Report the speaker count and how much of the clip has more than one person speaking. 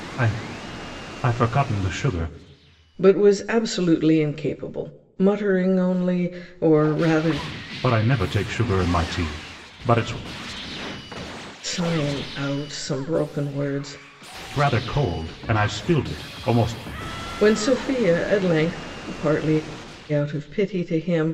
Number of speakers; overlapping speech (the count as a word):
two, no overlap